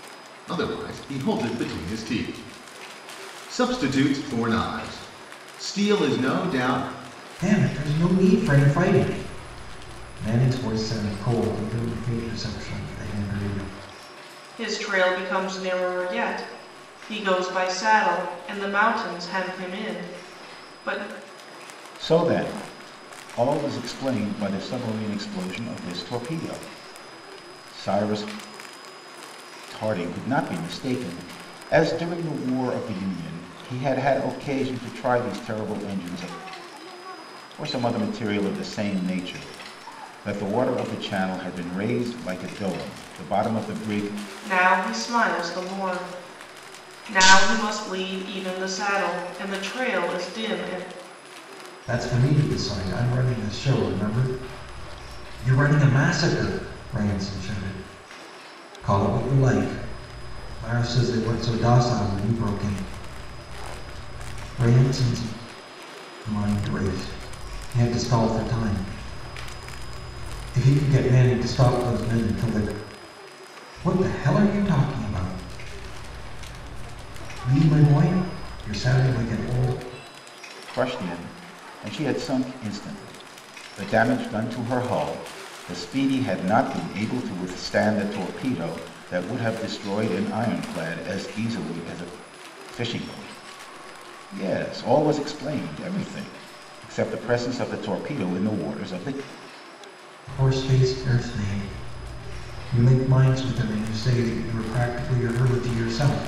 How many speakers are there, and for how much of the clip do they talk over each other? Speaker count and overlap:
four, no overlap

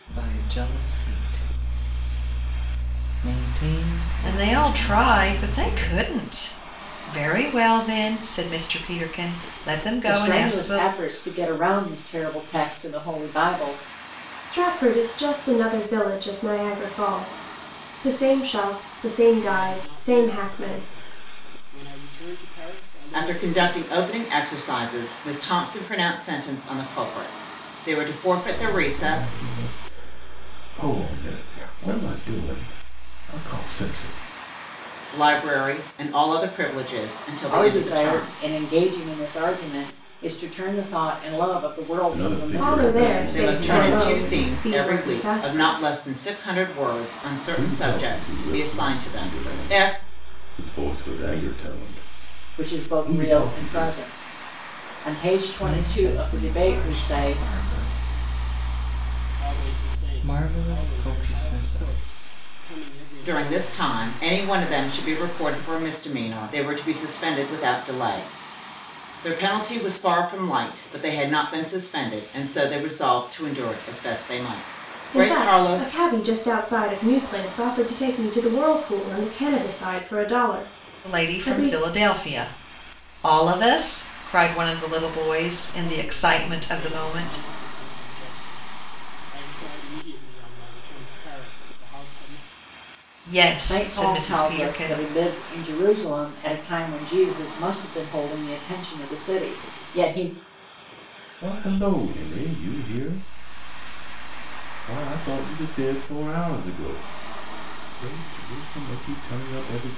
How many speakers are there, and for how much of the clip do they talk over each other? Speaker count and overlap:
seven, about 24%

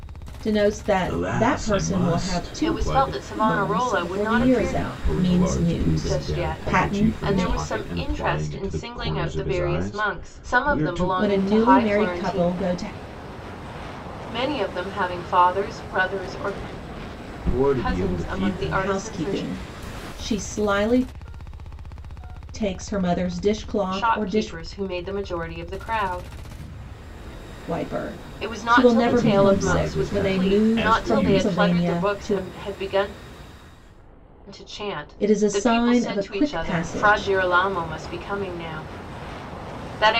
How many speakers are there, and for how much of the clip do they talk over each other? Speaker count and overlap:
three, about 50%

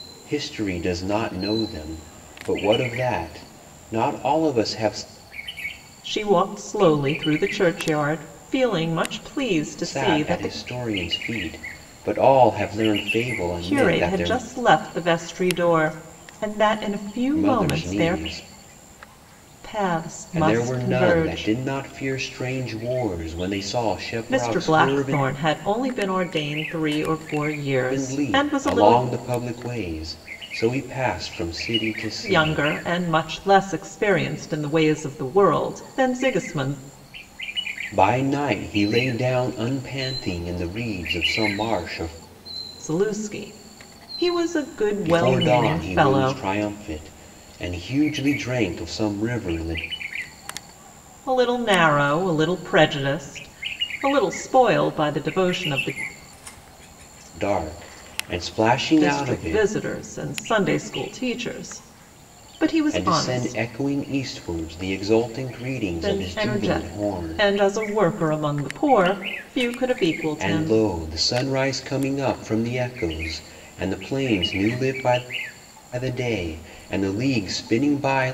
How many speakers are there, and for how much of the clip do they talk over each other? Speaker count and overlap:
two, about 14%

